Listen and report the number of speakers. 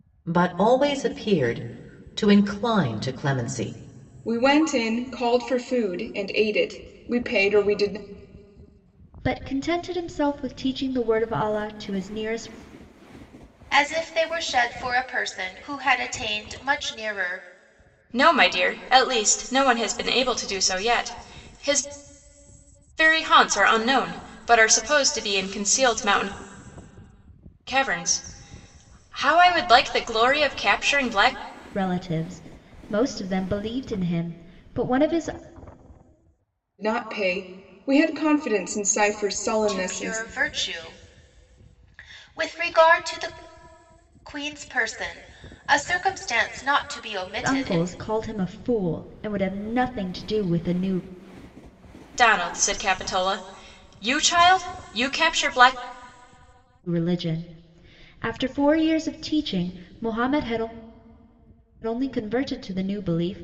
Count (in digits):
5